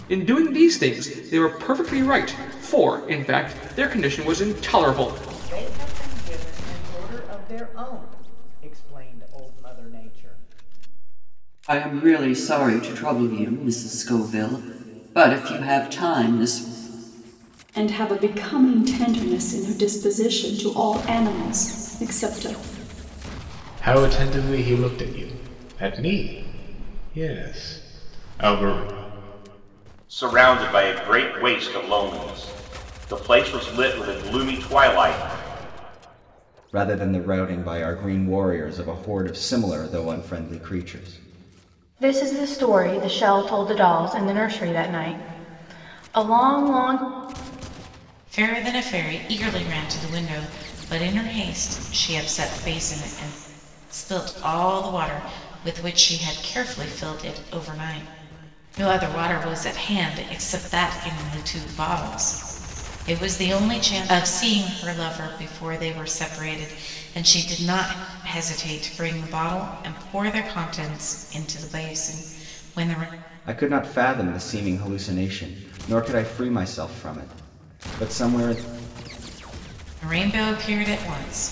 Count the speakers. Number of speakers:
9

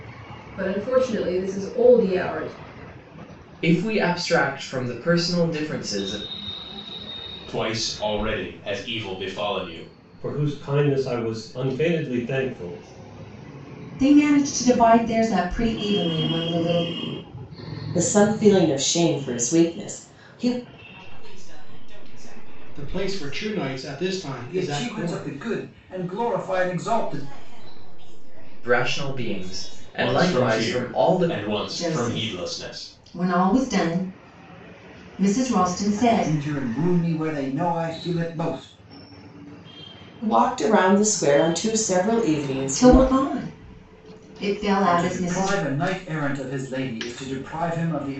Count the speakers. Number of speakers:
9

